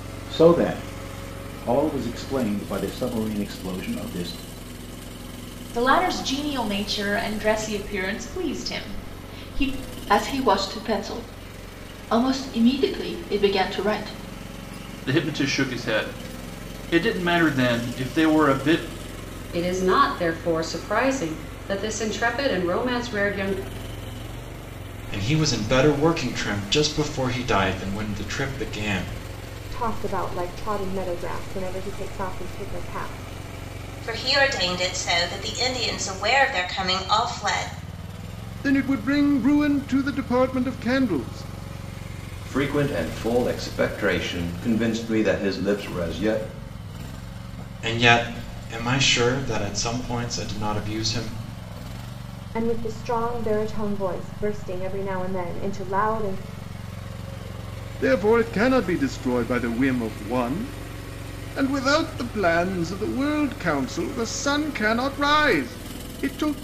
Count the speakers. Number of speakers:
ten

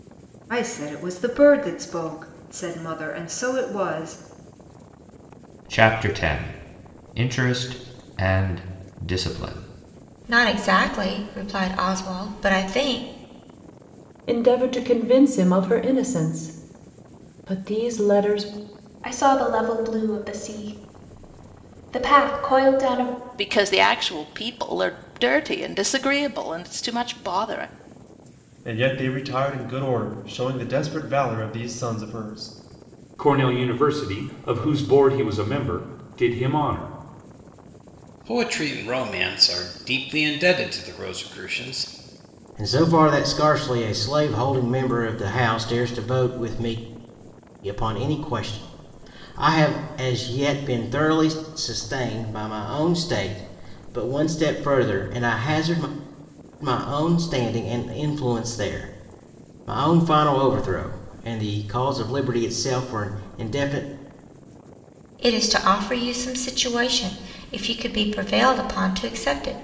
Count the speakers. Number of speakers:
ten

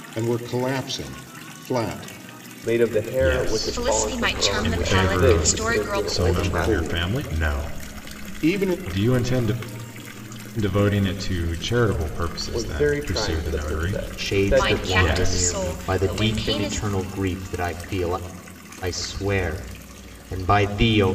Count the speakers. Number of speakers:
five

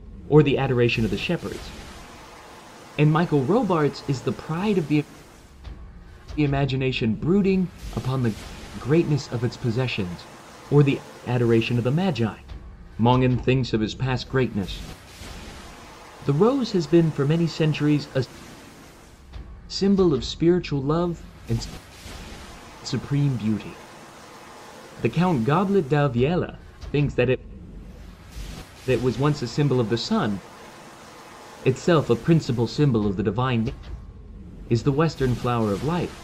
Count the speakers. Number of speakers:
one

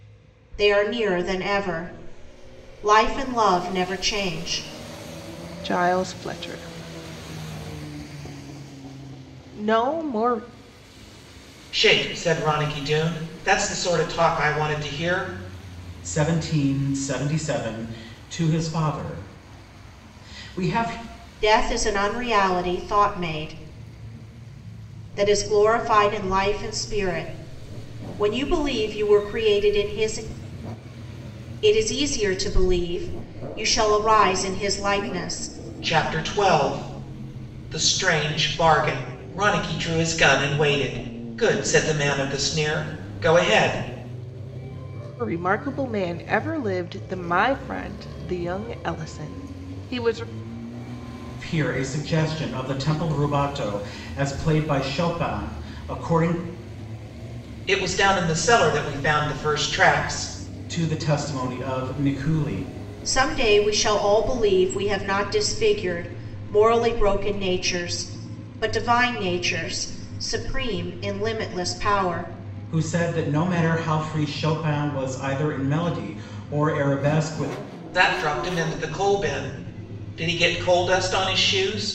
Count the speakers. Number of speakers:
four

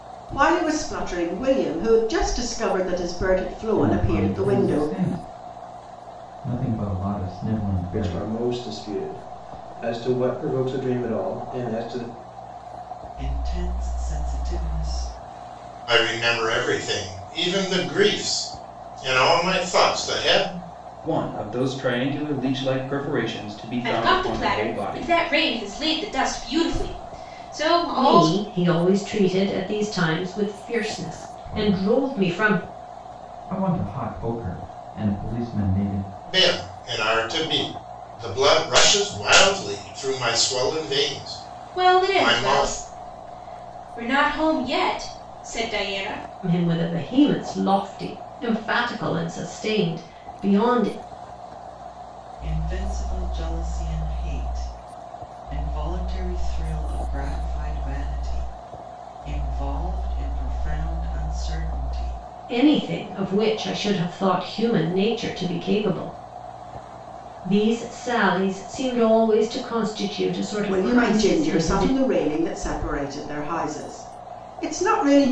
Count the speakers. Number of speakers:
eight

